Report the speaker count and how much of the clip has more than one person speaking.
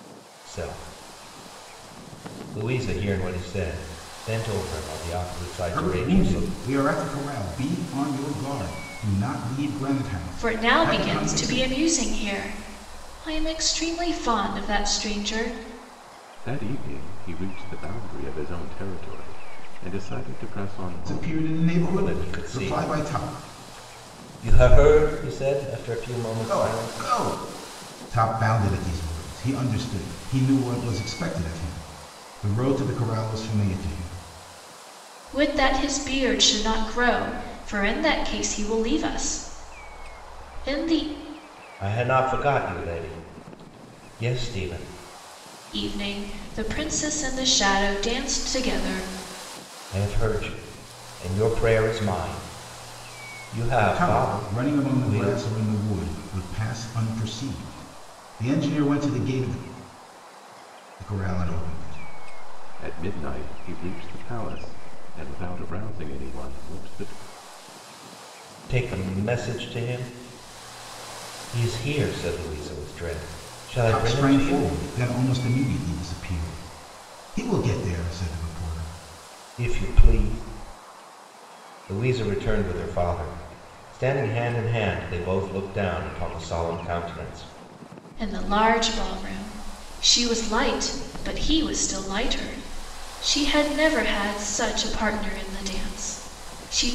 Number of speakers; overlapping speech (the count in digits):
4, about 9%